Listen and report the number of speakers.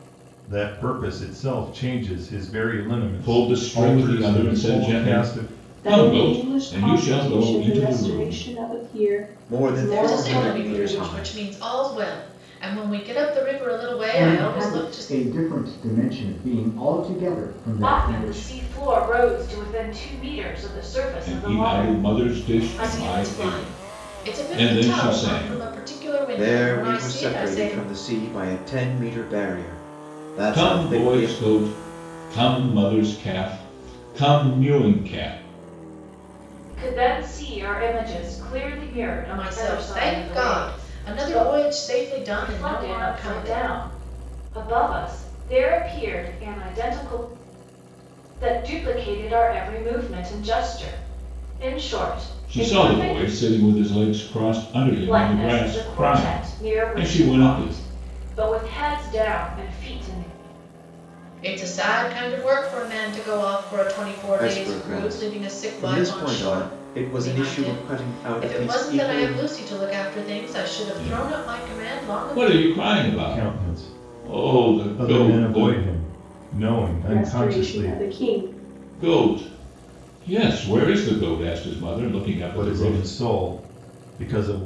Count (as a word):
seven